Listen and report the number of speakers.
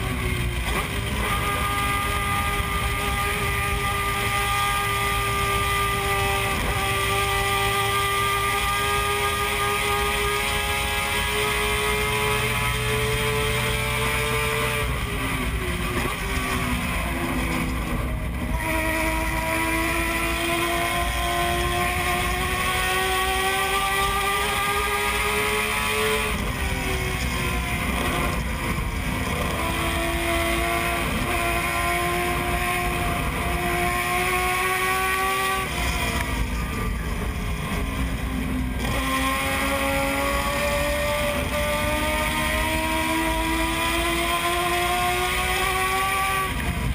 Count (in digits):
0